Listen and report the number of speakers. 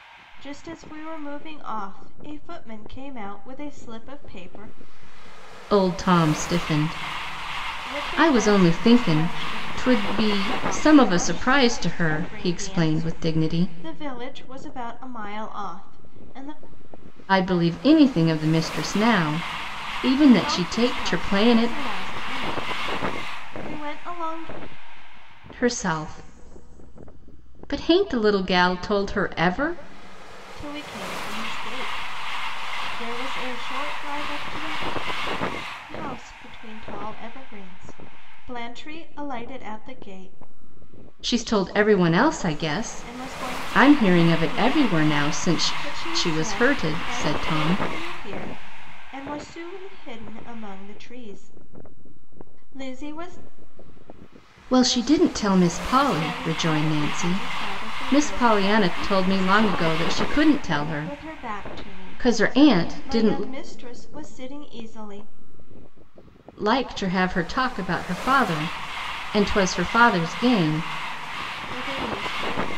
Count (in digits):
2